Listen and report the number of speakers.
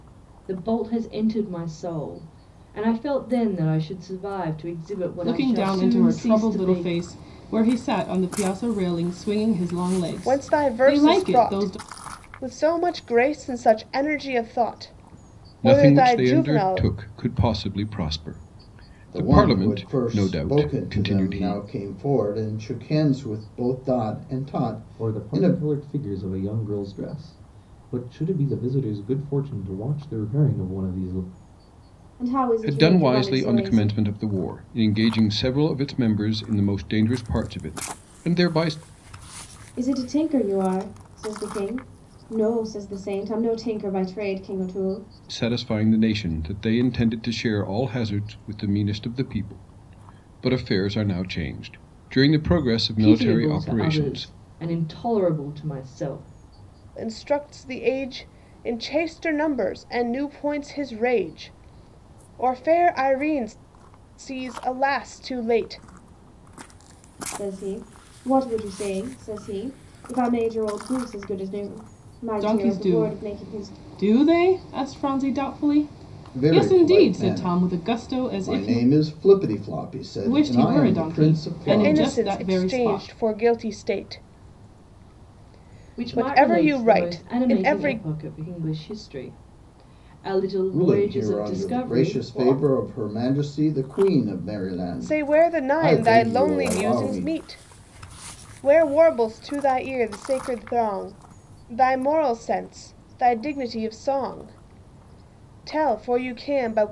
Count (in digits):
7